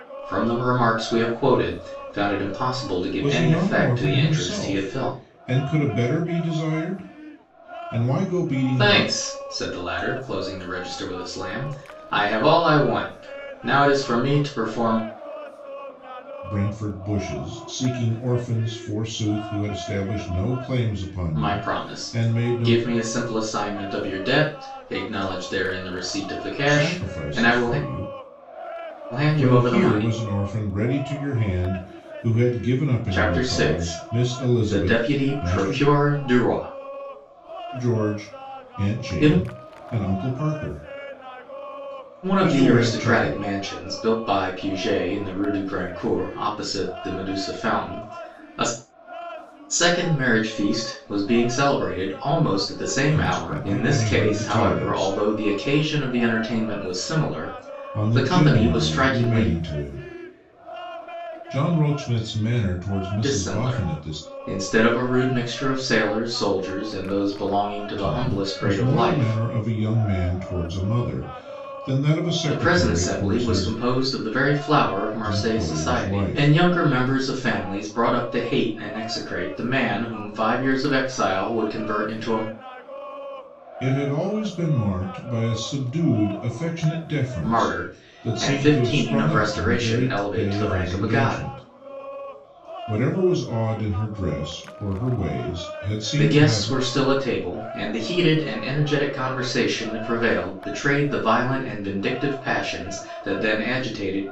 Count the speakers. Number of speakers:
two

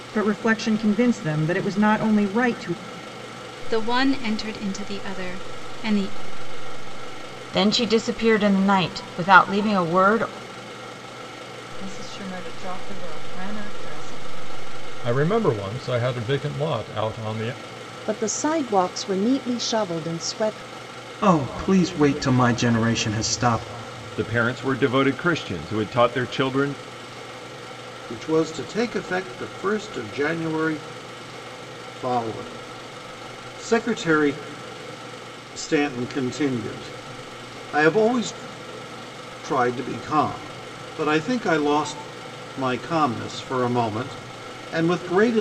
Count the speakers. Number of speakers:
nine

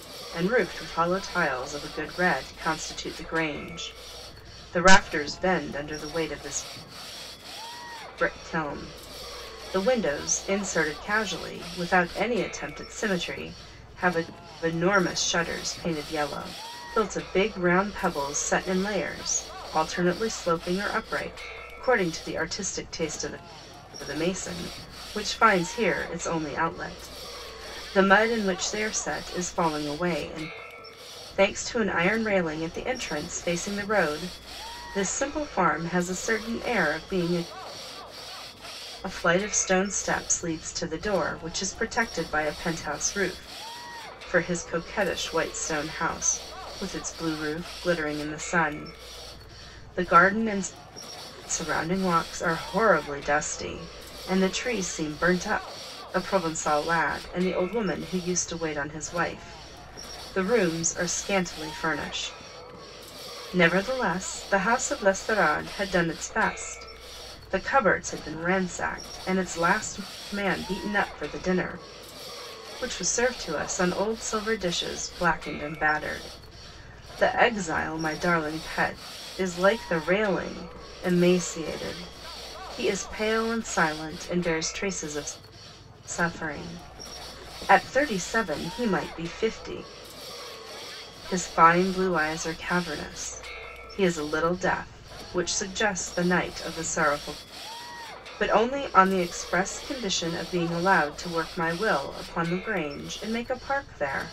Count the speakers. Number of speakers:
one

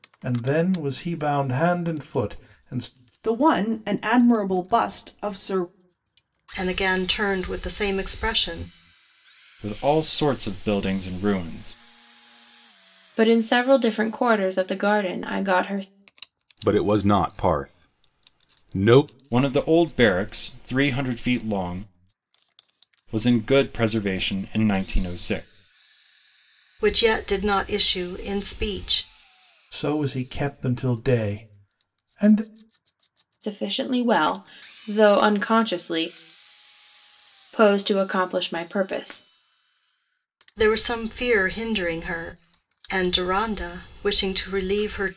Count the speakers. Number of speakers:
six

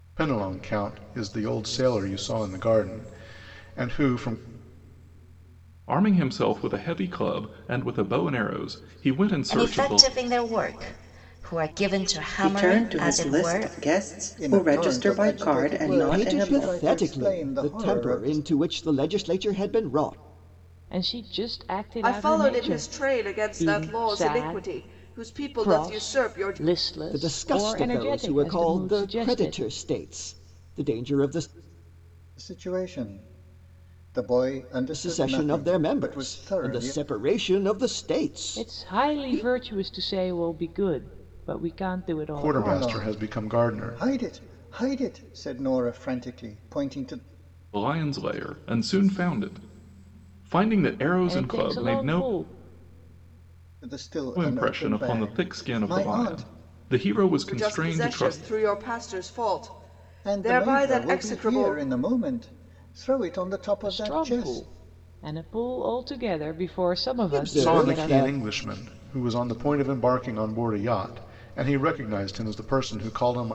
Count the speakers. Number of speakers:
eight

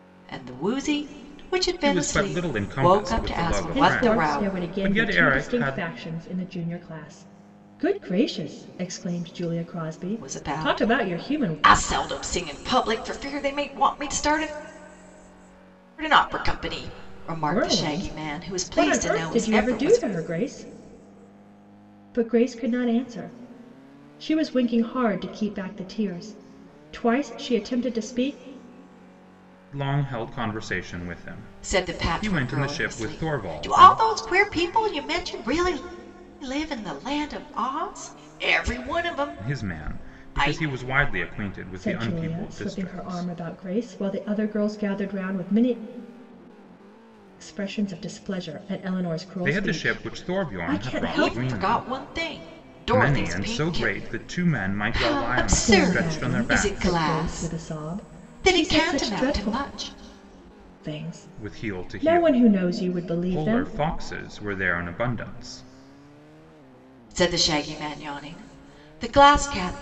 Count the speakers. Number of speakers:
three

